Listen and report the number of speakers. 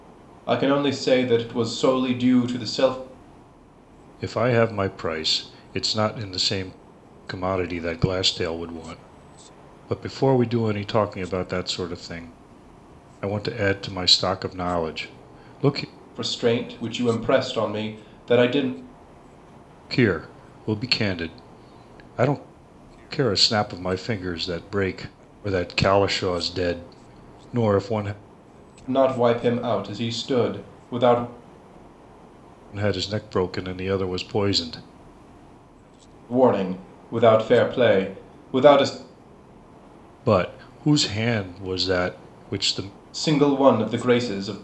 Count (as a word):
two